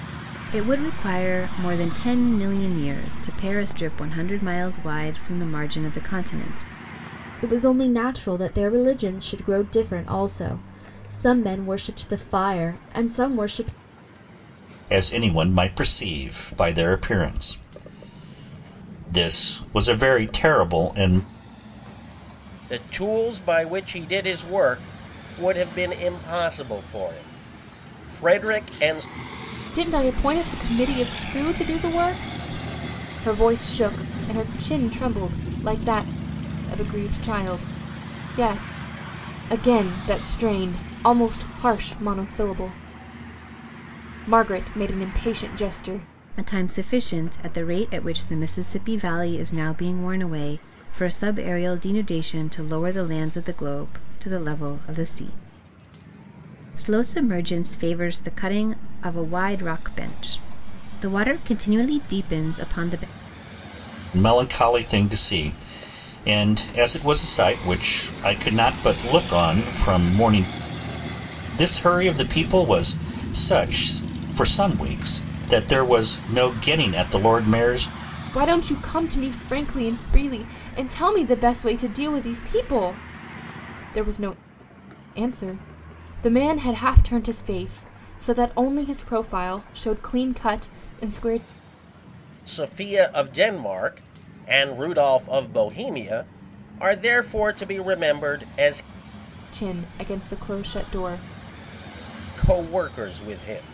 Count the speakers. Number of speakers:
five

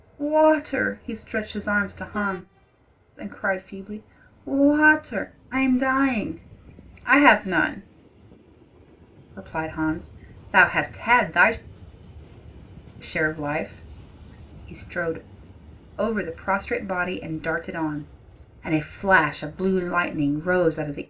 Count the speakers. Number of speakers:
one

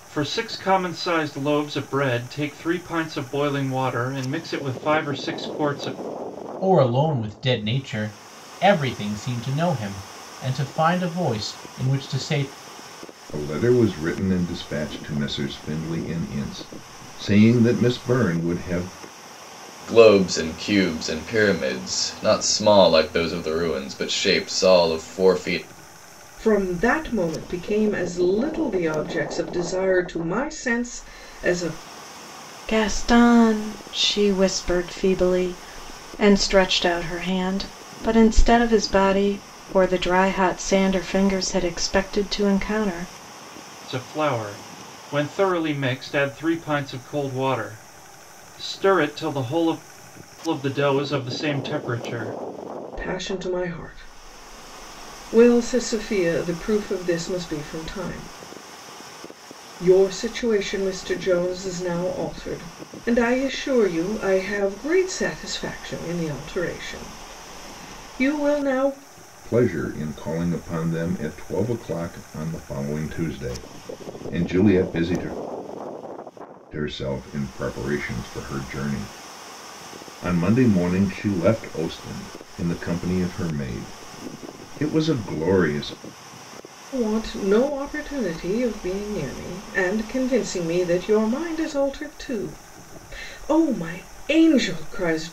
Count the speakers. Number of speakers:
six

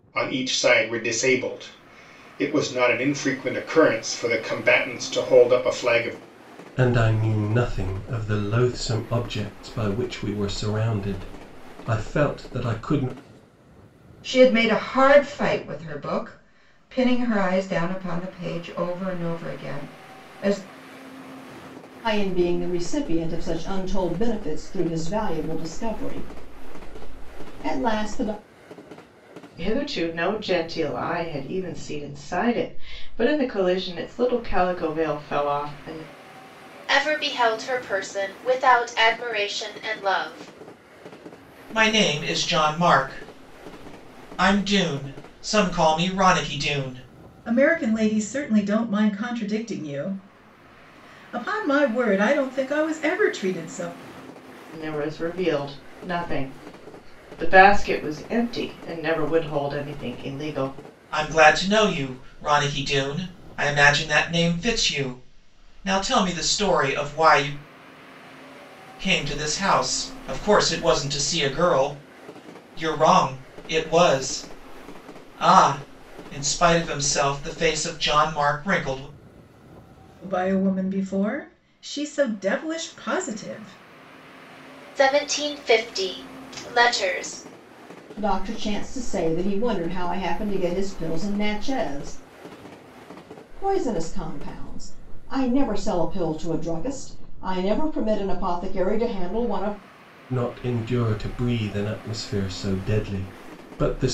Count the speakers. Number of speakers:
eight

